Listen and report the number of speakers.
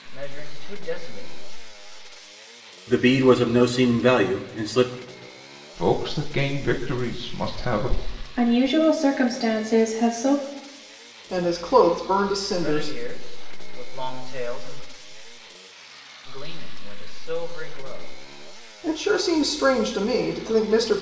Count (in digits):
5